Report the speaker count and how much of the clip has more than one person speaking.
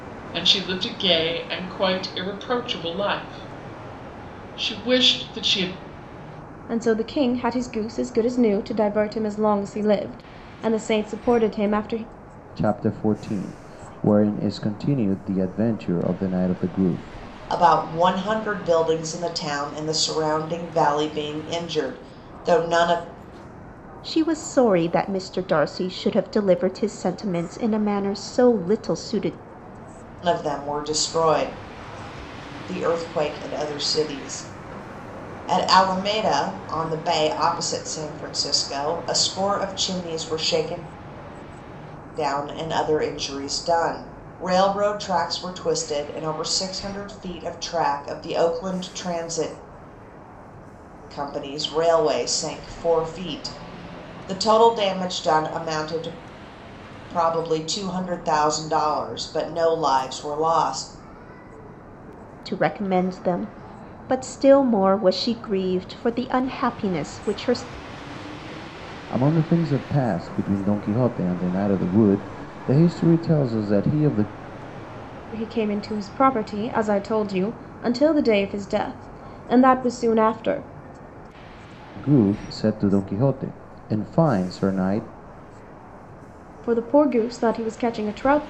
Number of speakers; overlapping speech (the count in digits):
5, no overlap